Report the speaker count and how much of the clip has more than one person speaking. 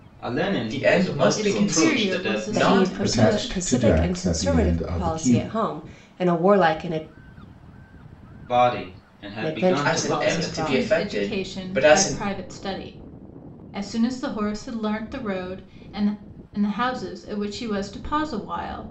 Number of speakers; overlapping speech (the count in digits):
5, about 40%